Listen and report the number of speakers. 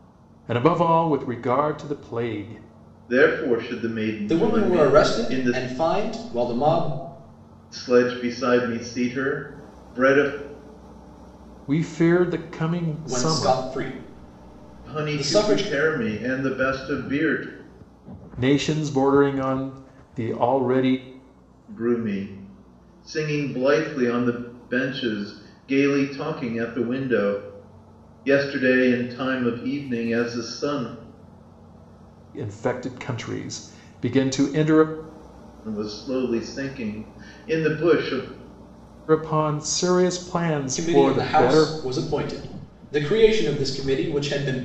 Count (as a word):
three